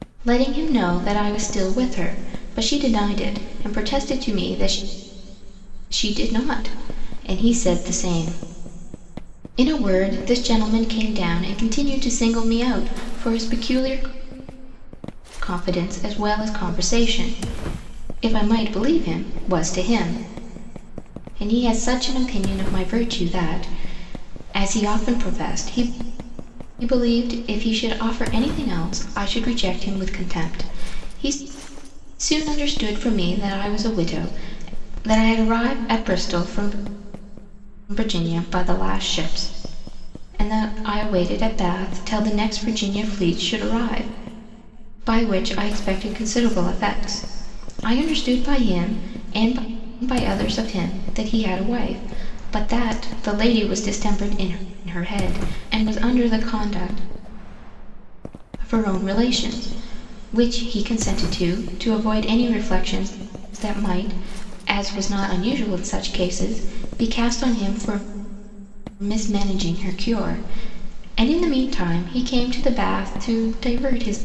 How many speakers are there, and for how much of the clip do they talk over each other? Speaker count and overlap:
one, no overlap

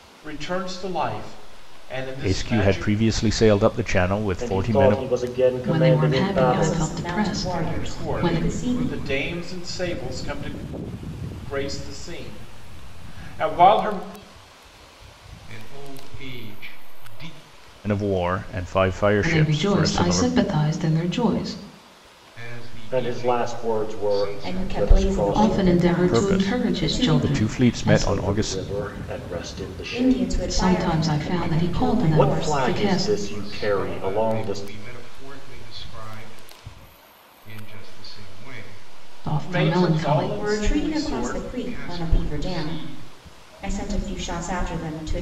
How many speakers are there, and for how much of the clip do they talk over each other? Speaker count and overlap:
six, about 44%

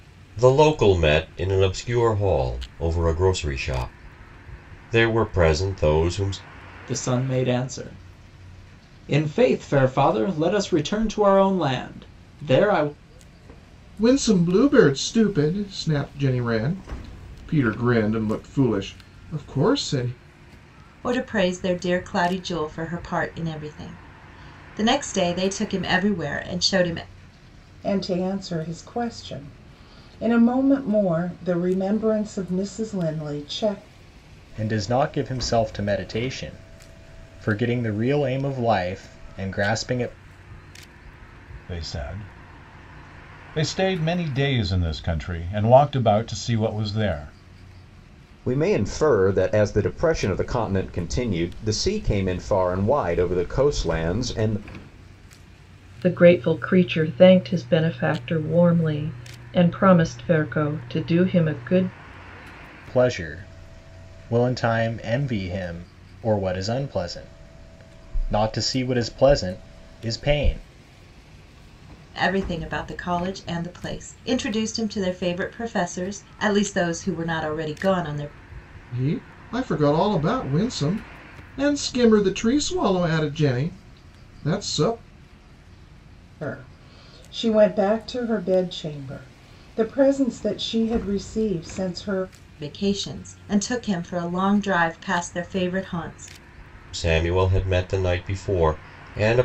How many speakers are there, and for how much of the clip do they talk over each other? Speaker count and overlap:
nine, no overlap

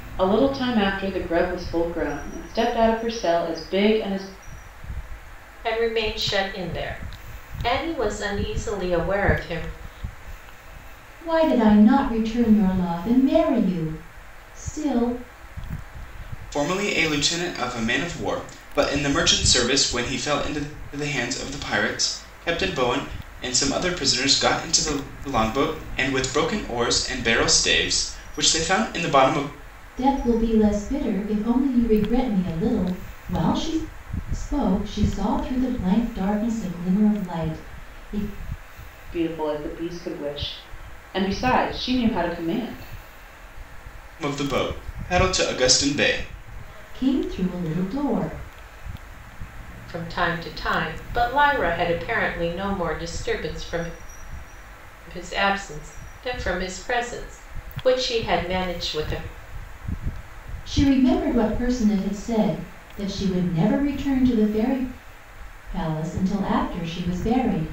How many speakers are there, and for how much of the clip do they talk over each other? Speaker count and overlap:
four, no overlap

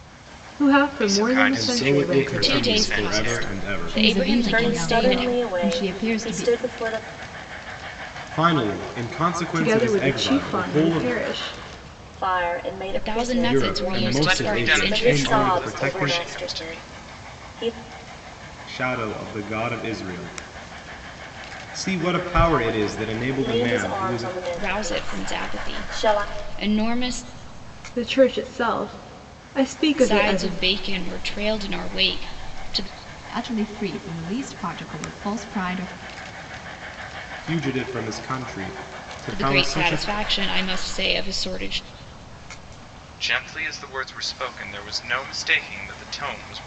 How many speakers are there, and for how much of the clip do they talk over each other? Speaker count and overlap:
six, about 33%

